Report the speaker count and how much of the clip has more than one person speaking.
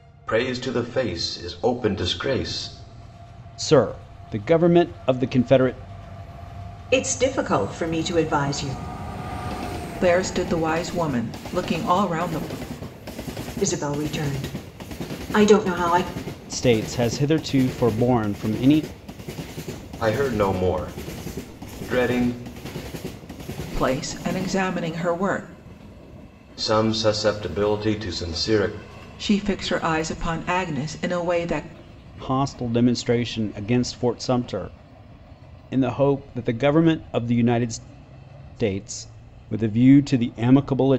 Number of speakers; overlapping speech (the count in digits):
4, no overlap